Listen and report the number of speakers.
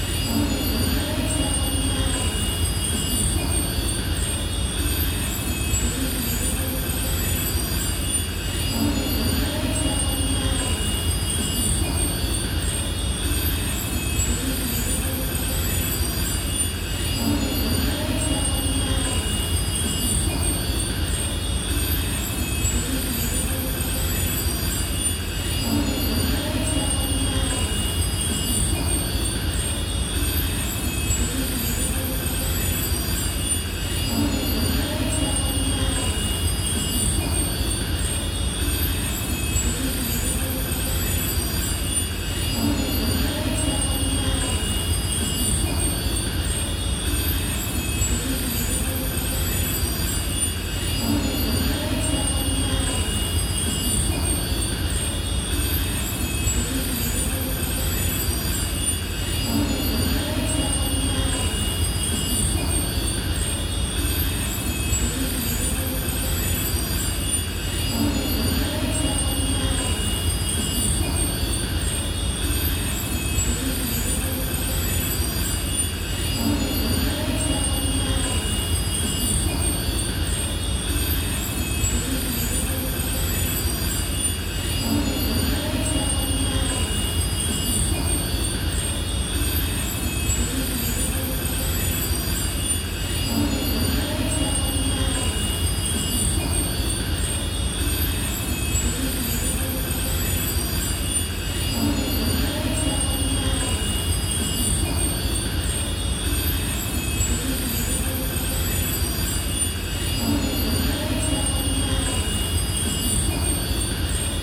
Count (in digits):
0